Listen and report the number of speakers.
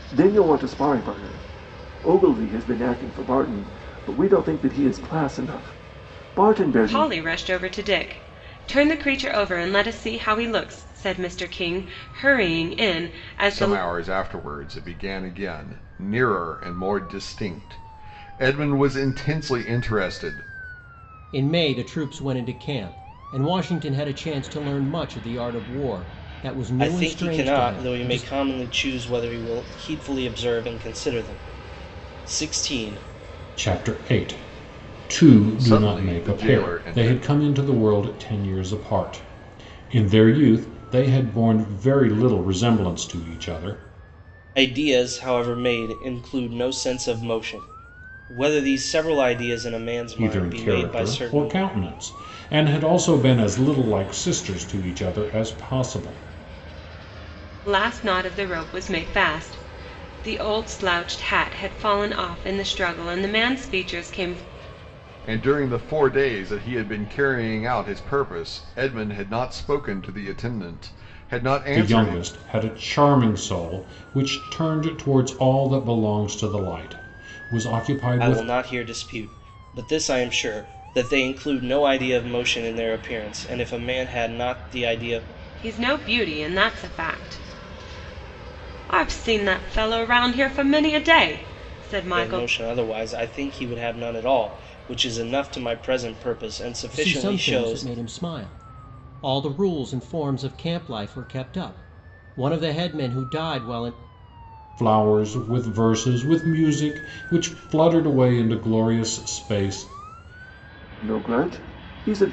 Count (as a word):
six